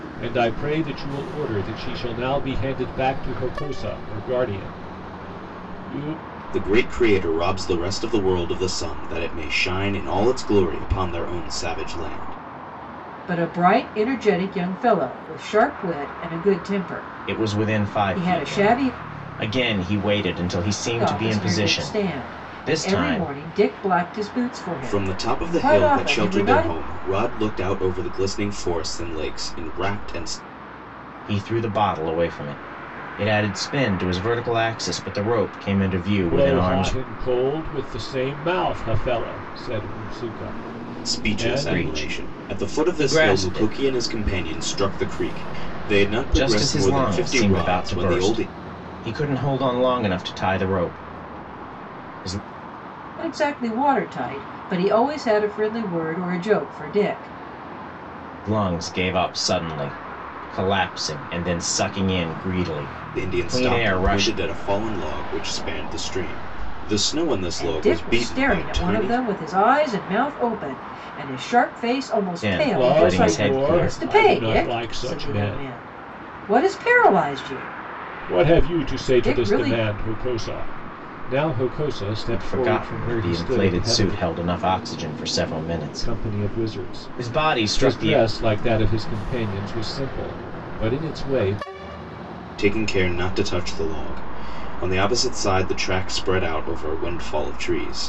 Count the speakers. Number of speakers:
4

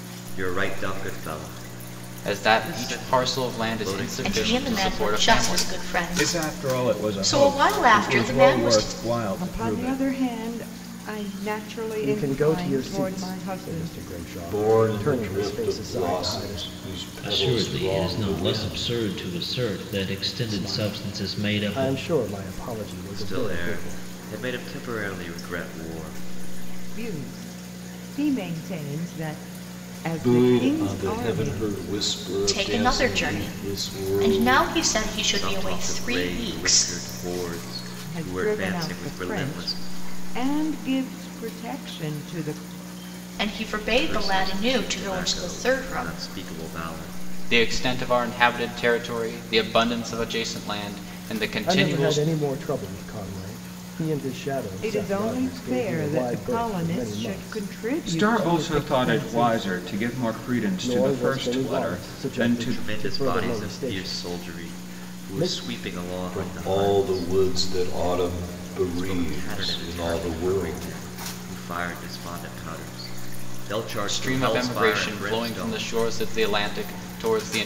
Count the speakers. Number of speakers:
8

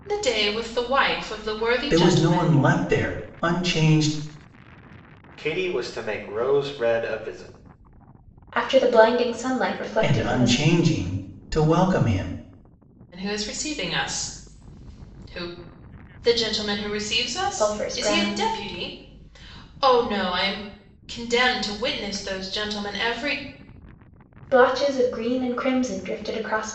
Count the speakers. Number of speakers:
4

